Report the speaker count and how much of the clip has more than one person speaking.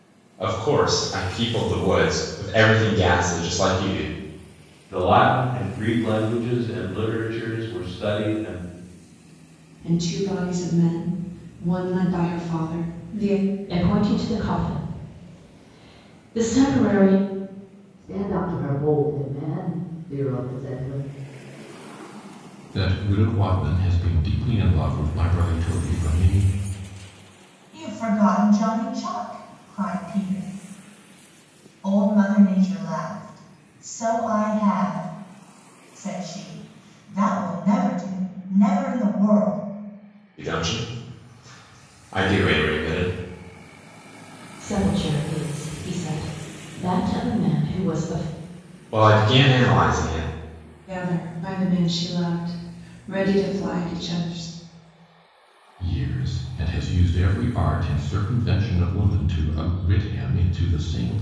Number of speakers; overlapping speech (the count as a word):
seven, no overlap